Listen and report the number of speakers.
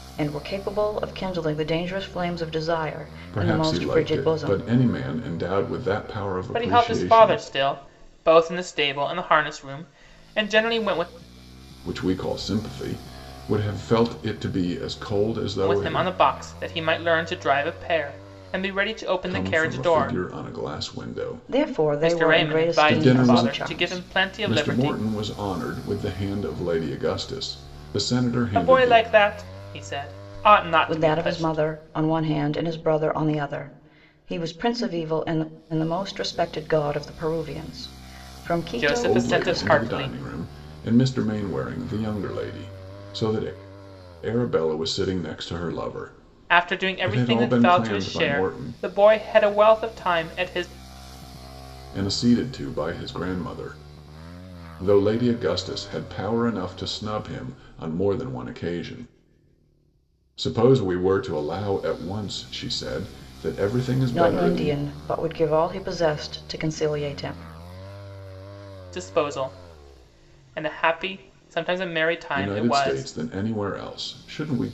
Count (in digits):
3